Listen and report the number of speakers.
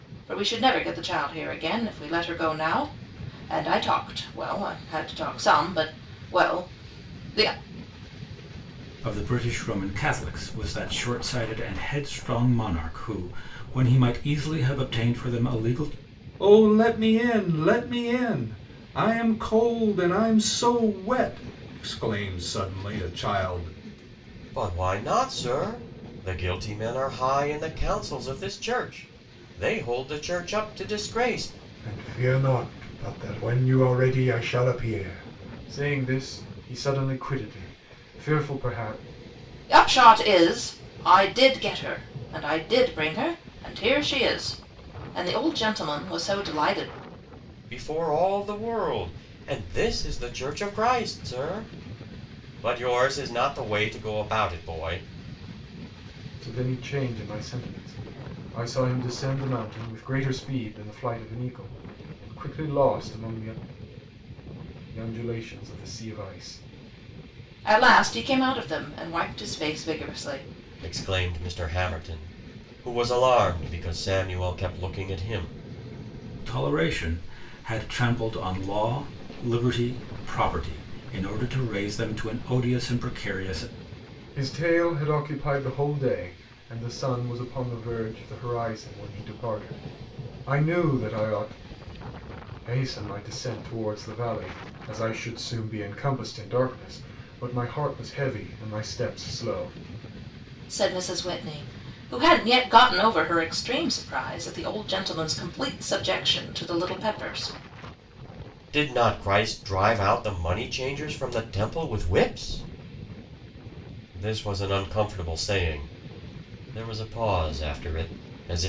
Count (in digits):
5